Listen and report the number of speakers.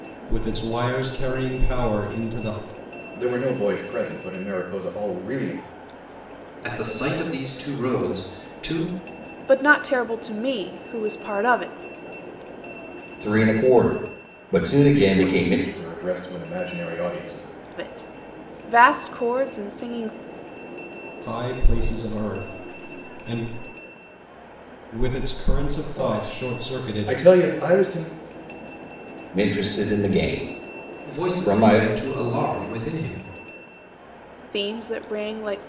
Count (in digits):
5